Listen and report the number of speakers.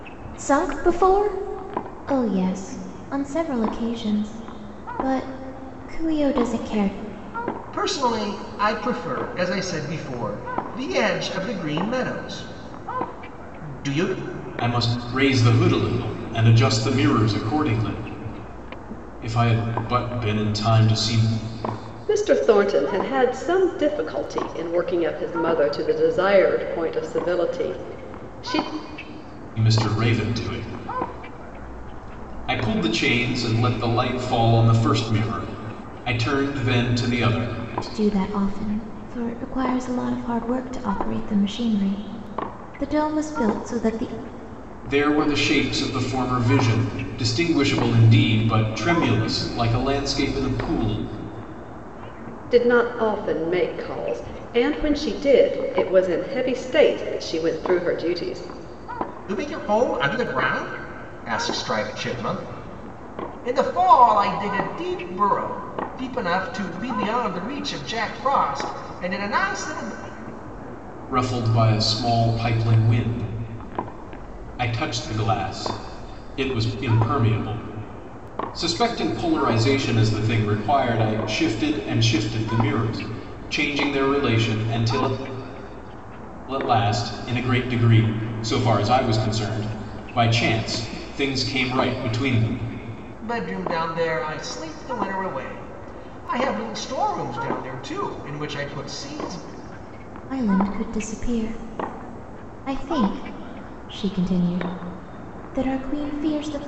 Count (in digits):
4